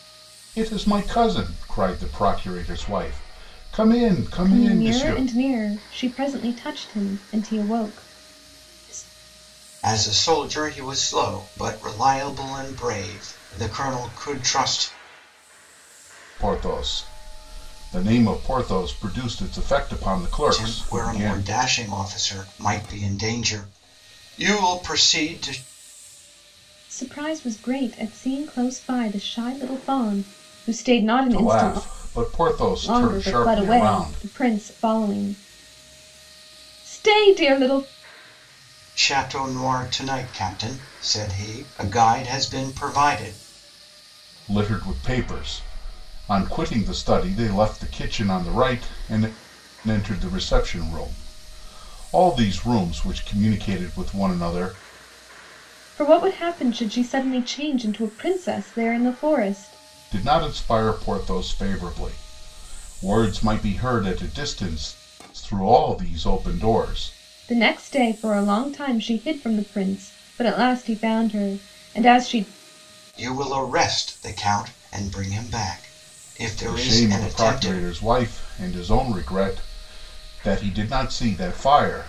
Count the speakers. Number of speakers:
3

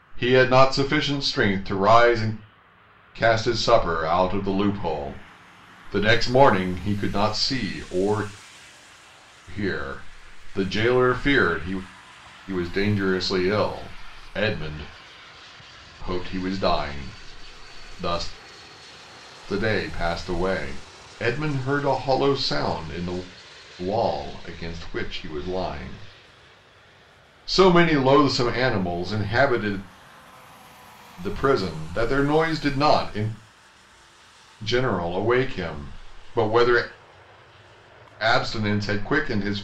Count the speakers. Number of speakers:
1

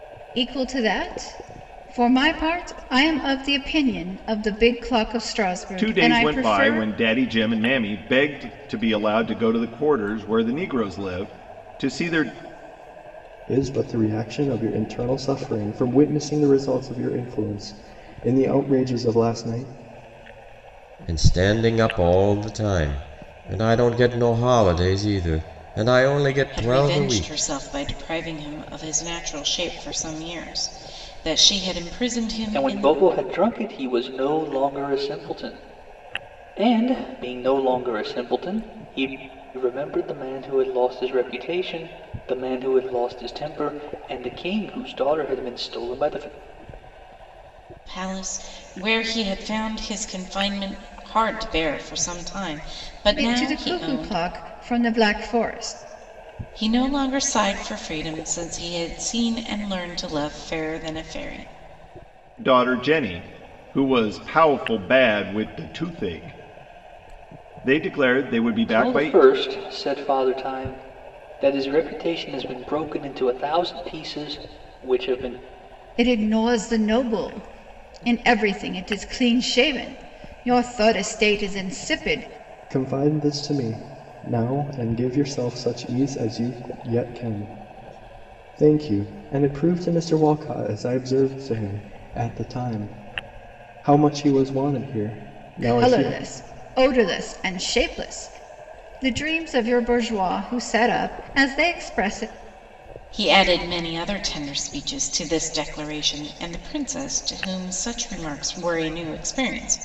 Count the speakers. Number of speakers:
6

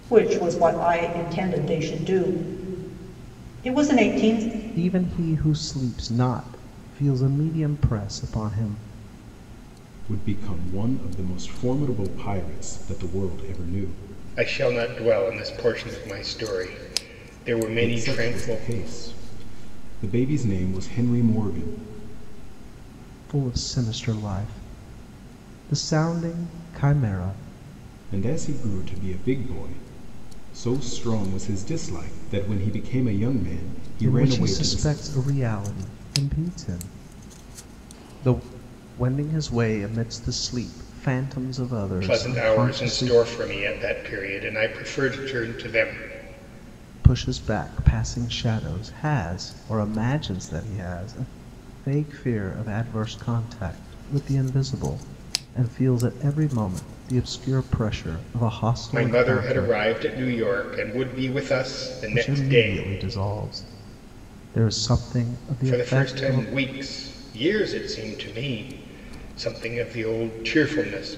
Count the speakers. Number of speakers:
4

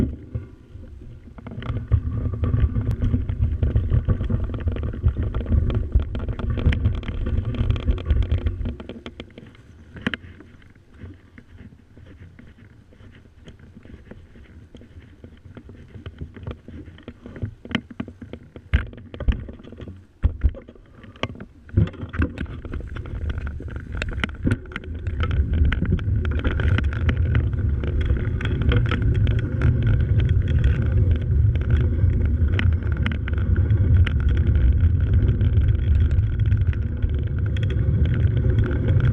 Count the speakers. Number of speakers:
0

